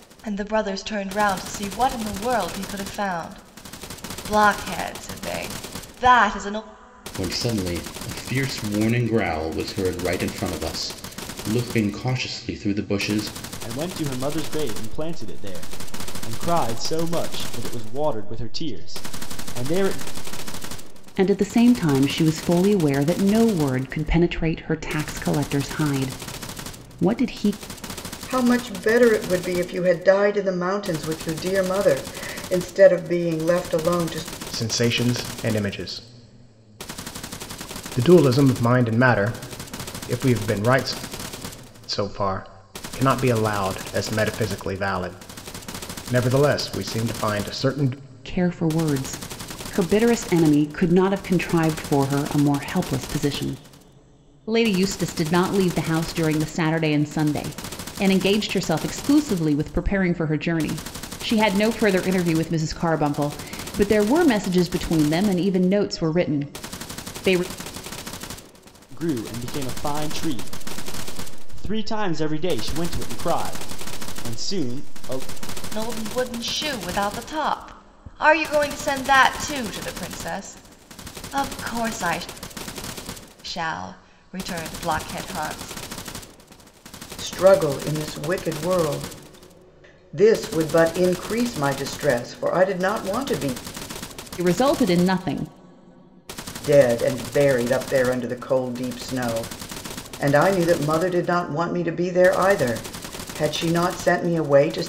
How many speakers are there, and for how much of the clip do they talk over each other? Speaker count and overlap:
6, no overlap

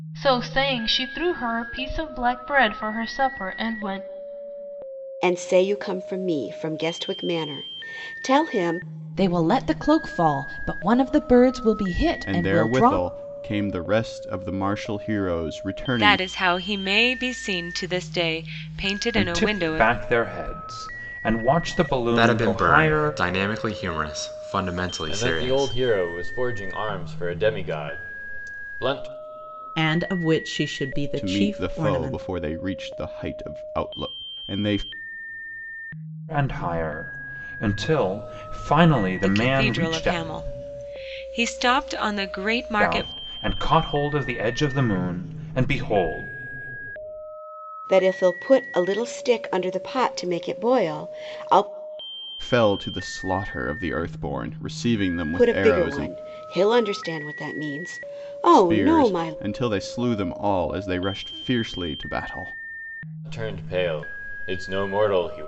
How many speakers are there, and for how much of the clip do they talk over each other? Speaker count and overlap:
9, about 13%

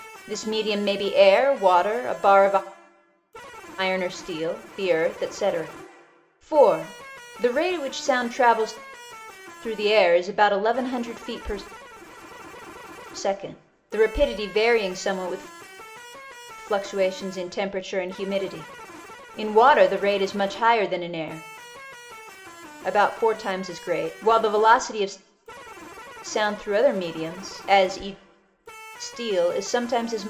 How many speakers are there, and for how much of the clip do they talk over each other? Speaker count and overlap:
1, no overlap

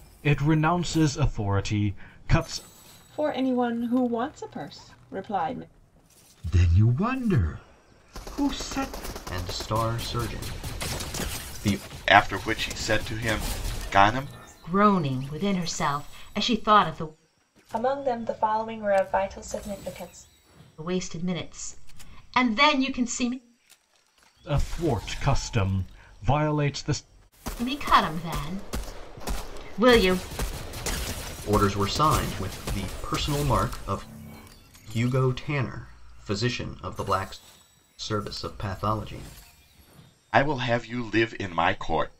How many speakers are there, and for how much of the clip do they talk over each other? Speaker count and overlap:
7, no overlap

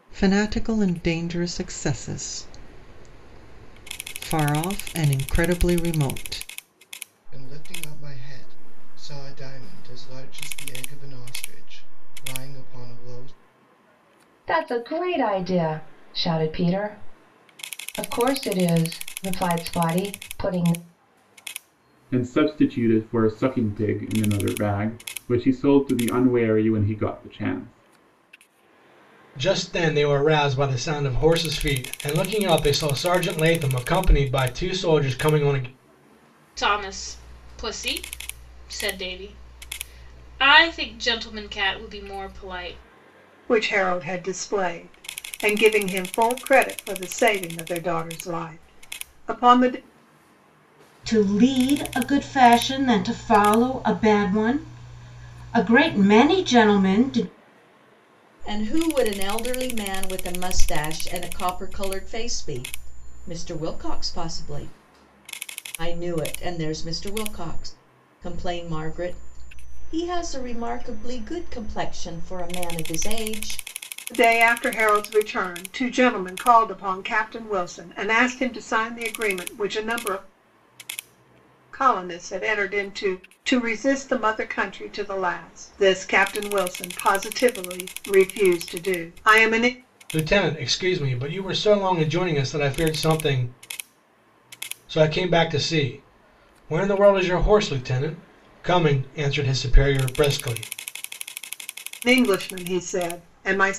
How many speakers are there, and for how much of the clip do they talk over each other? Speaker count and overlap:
9, no overlap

